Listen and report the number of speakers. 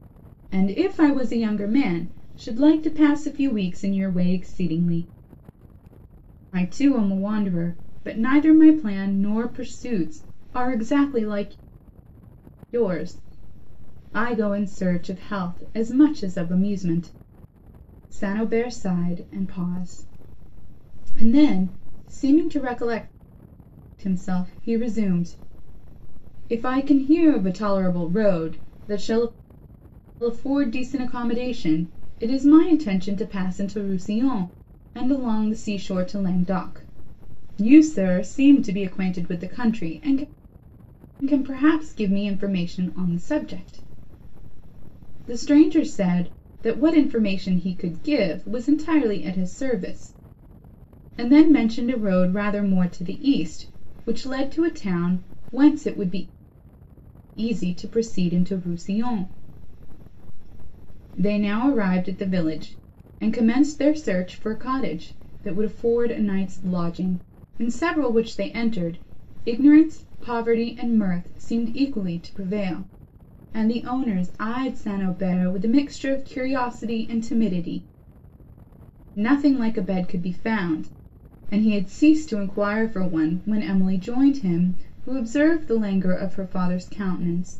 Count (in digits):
1